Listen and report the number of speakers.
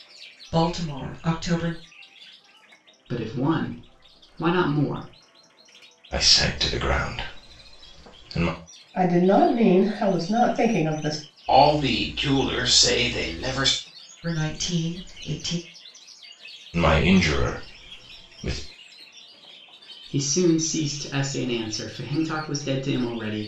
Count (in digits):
5